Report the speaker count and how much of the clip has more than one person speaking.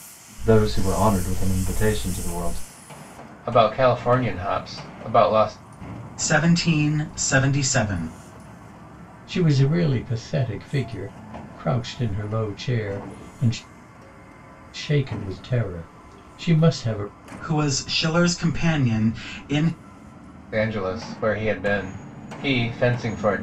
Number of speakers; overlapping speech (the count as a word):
four, no overlap